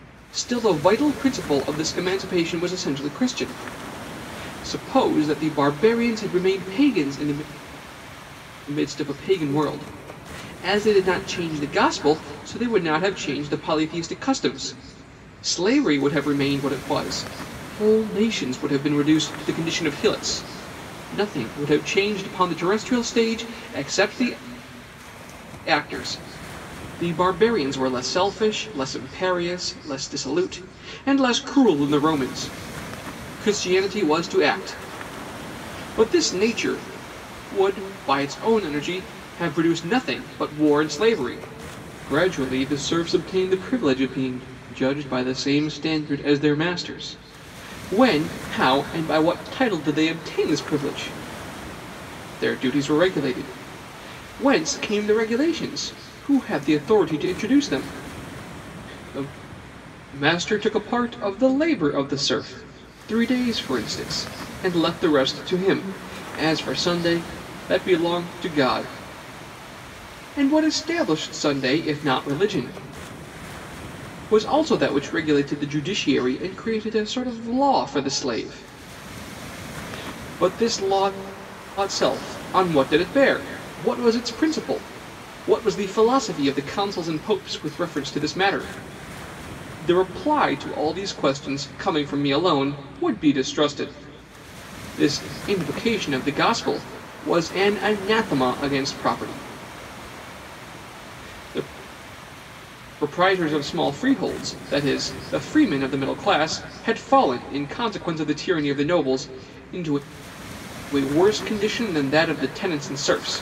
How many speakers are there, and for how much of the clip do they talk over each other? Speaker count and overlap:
one, no overlap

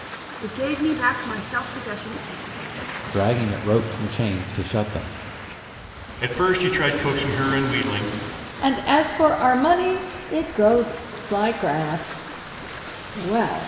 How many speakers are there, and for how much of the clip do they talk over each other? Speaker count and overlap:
four, no overlap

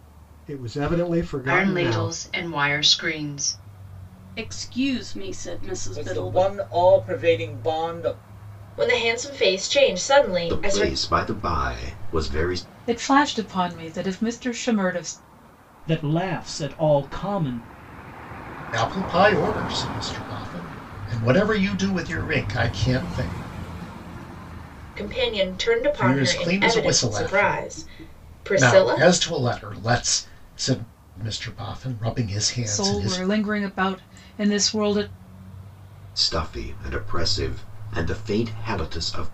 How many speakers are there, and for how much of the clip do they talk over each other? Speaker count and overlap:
nine, about 12%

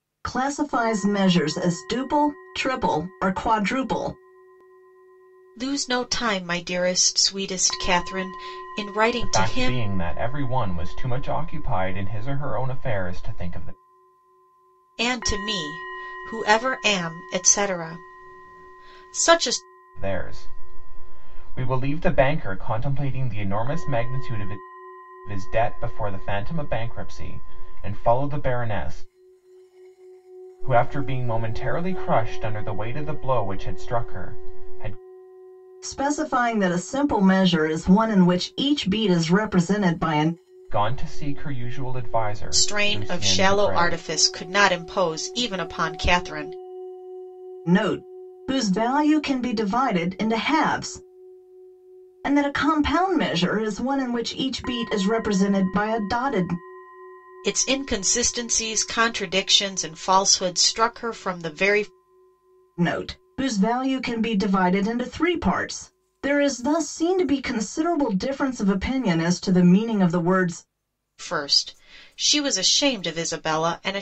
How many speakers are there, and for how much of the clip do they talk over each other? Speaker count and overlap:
three, about 3%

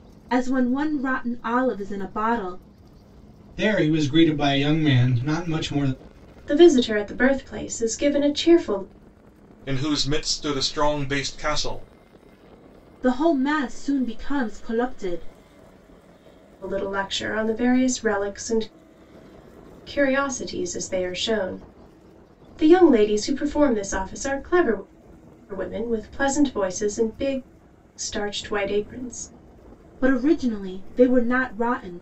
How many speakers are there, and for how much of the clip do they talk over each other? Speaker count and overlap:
four, no overlap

